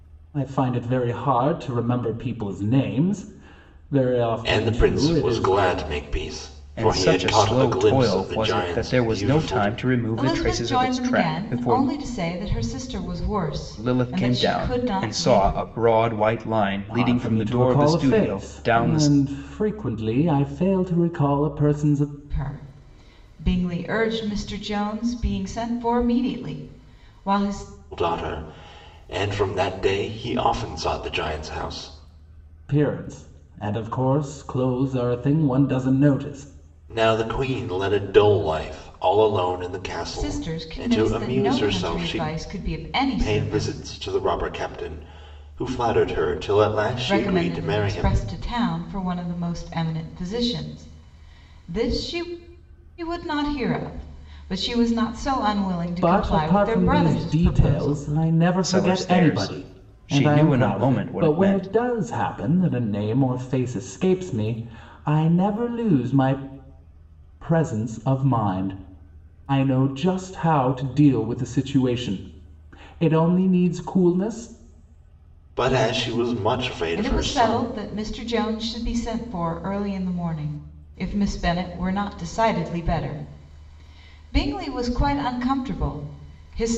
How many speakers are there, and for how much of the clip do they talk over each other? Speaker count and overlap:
4, about 23%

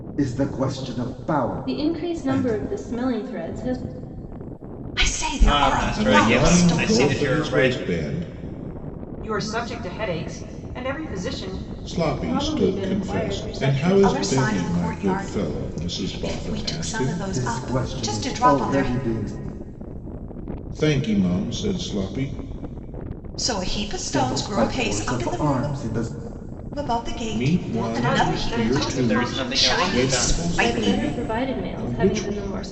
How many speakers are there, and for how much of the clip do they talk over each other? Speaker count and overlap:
6, about 51%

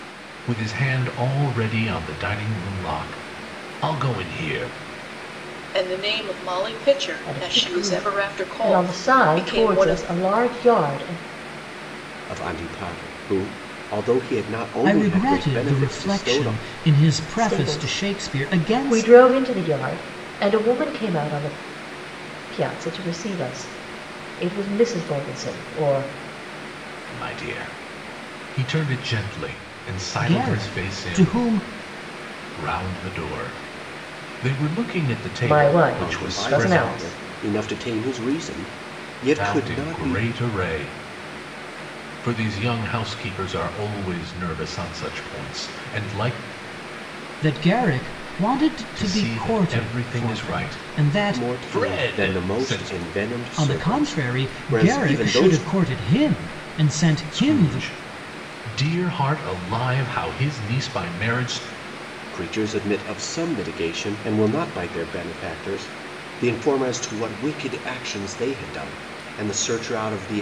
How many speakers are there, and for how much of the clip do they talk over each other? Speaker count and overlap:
5, about 24%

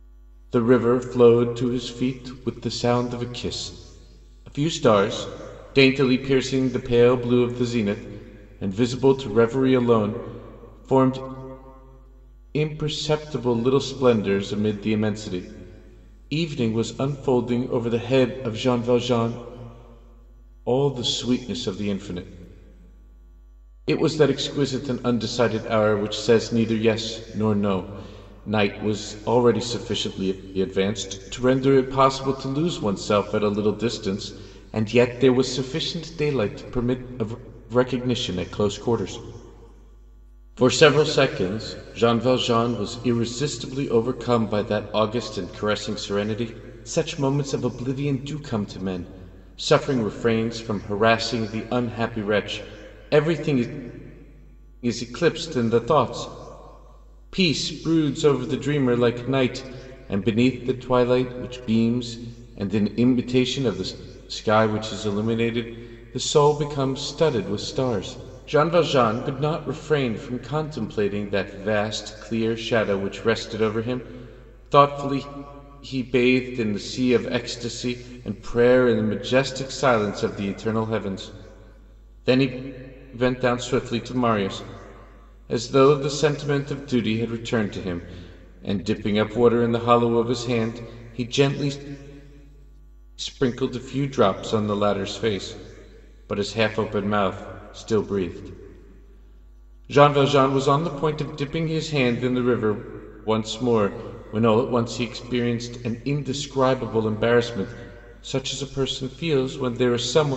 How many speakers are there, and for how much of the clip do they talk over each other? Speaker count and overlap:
1, no overlap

